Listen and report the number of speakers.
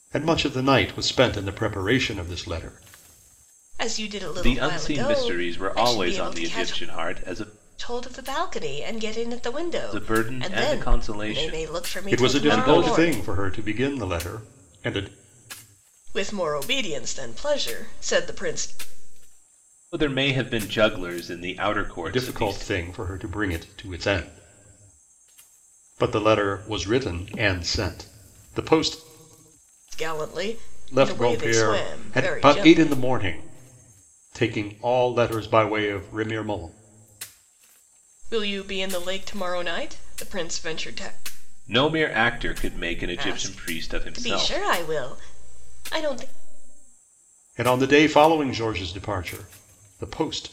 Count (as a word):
three